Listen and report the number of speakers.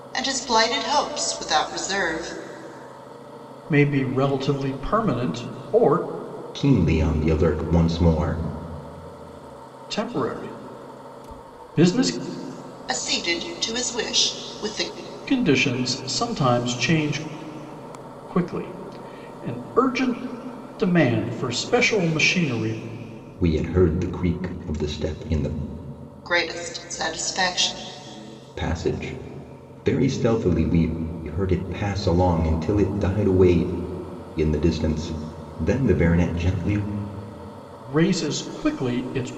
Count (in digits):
3